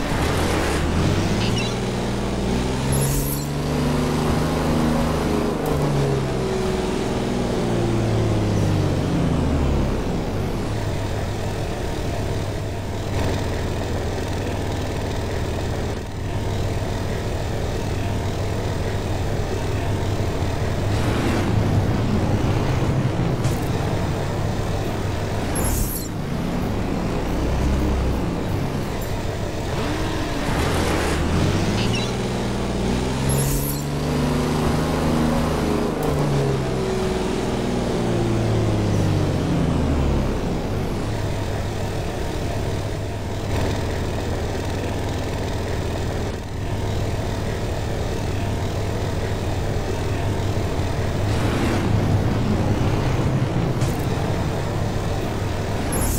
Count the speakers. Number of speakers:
zero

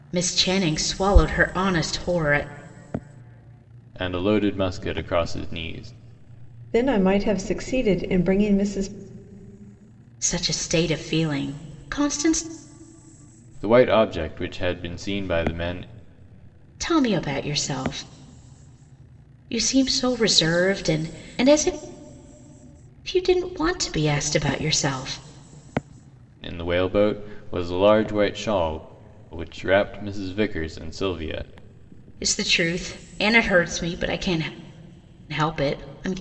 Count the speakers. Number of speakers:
three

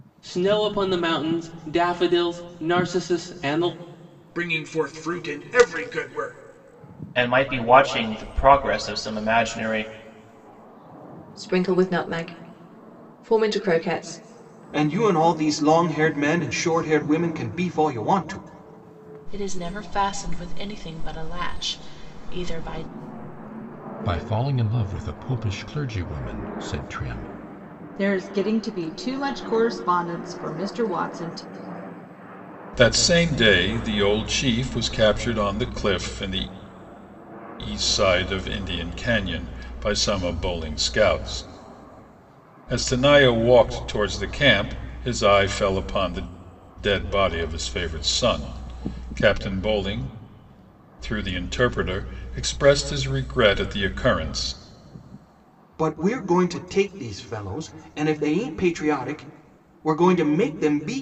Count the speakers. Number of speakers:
nine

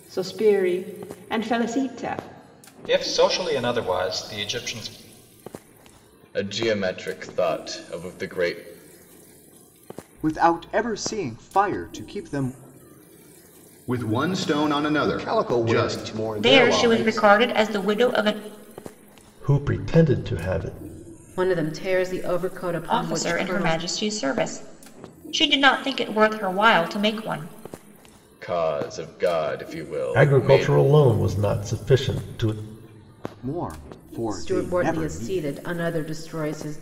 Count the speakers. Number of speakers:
nine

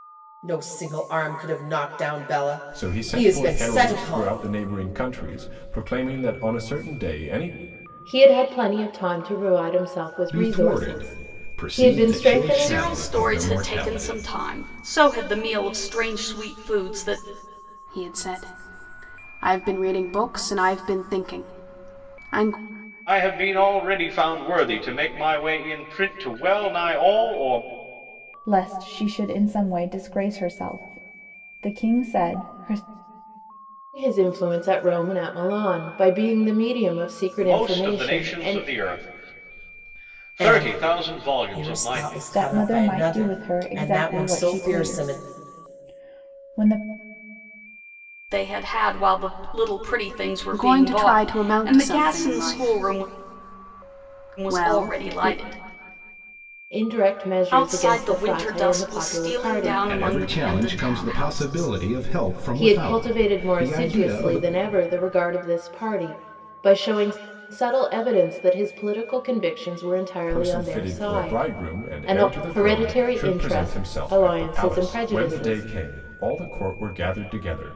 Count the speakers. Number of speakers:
eight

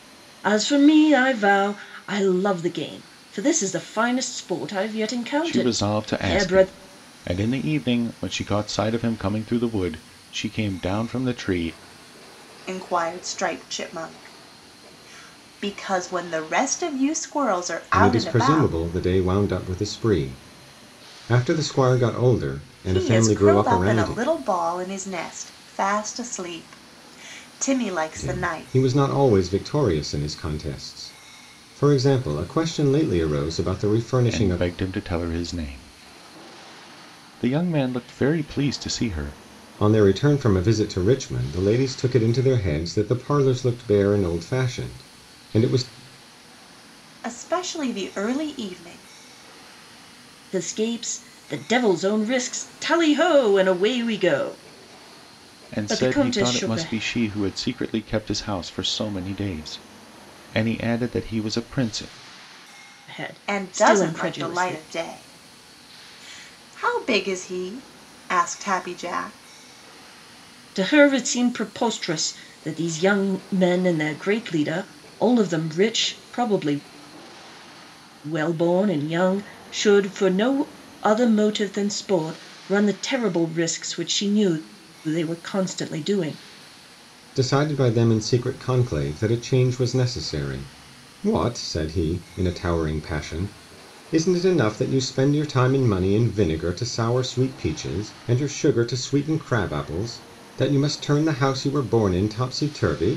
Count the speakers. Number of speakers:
four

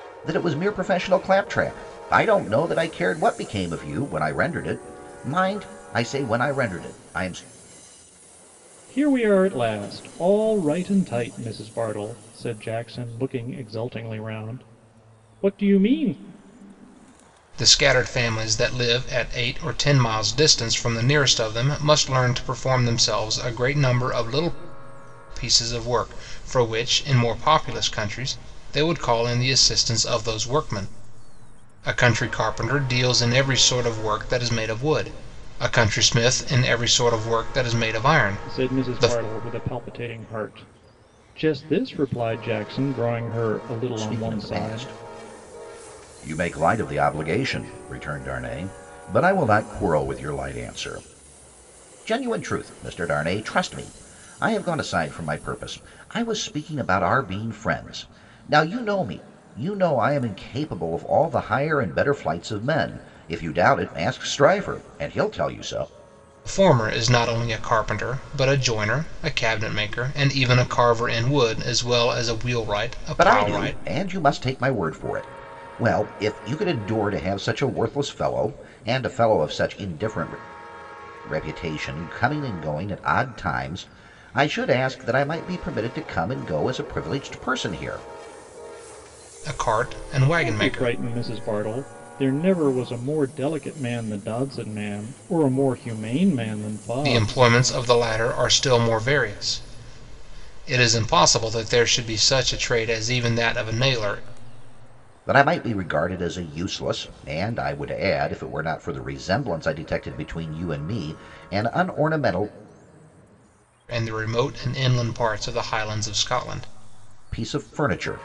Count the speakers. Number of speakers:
three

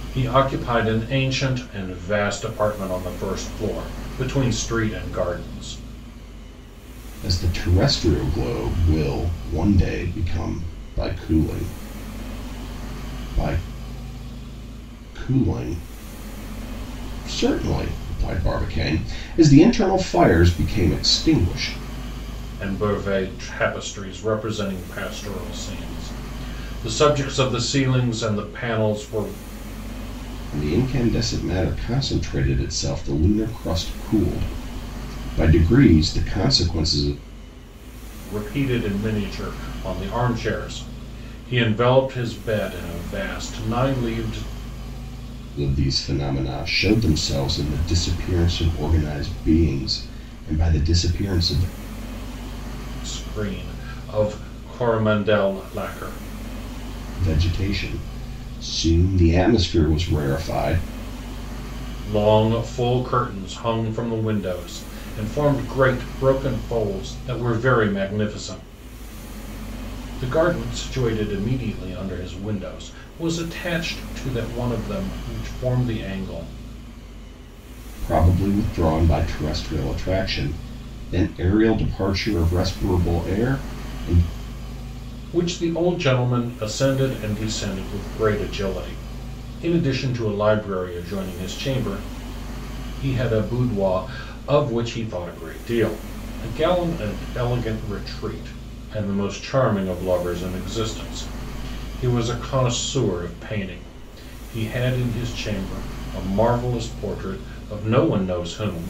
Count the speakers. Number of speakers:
two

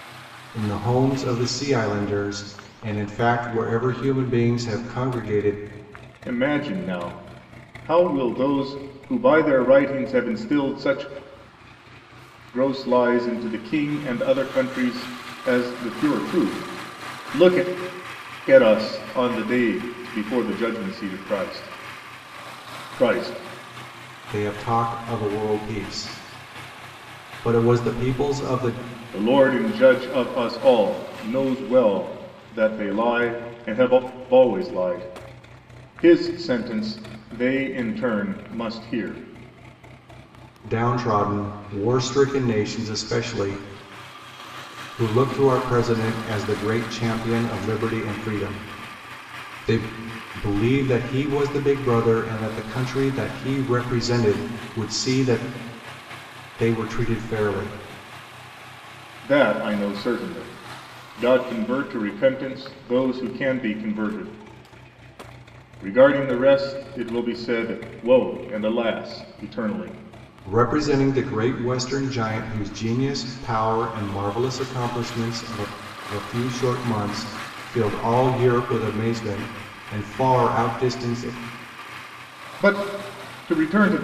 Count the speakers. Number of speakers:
two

